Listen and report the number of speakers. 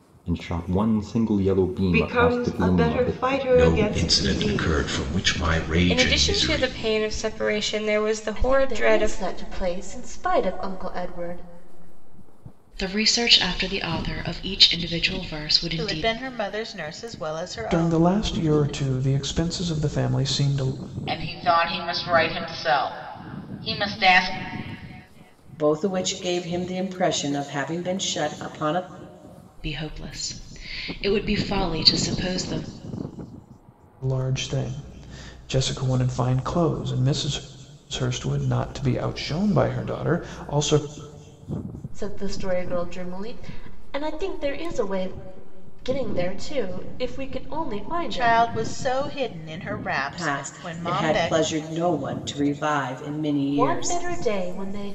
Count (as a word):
ten